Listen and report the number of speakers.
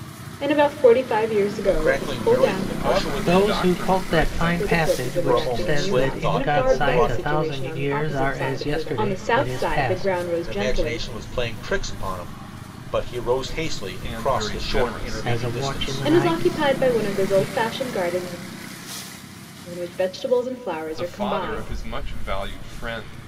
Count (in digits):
4